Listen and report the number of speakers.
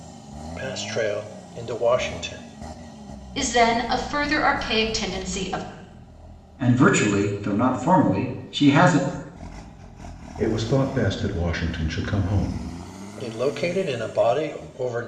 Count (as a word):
four